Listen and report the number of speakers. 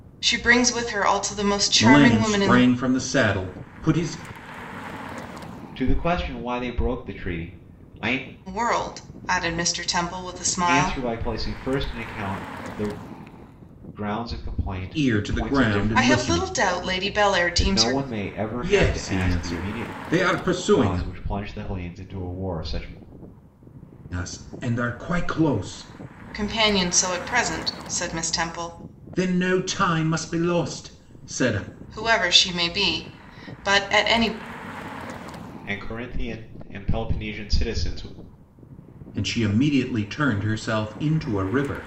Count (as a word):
three